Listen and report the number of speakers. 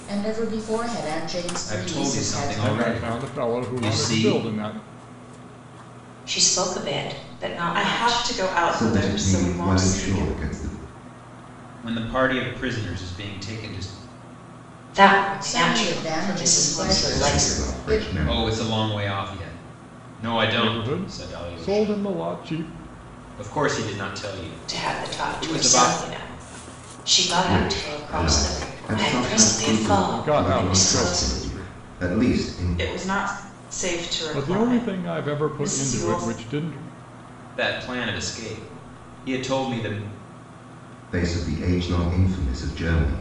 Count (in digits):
6